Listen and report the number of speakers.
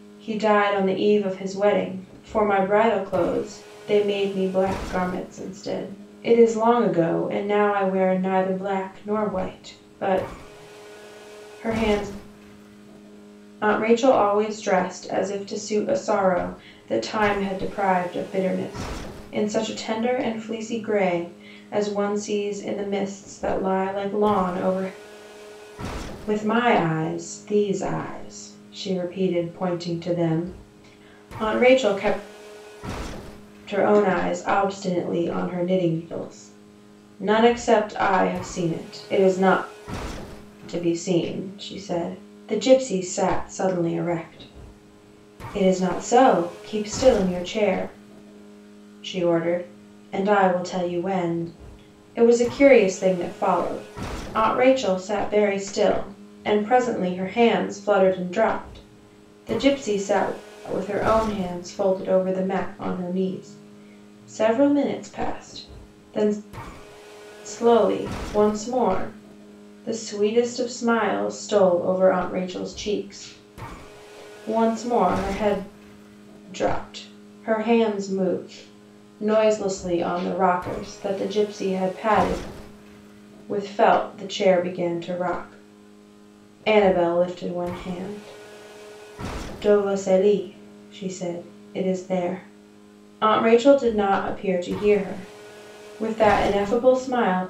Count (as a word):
one